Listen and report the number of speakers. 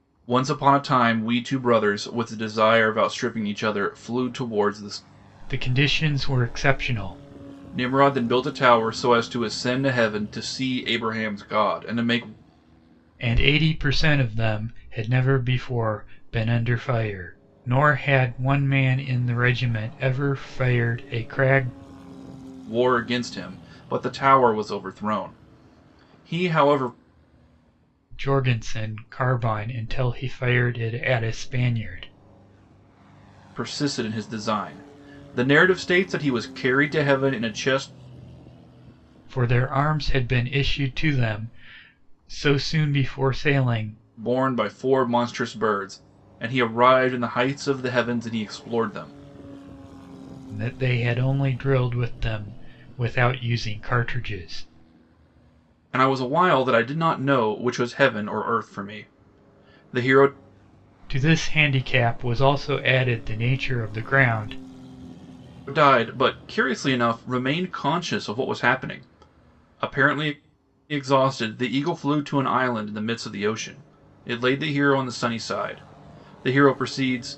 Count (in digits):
2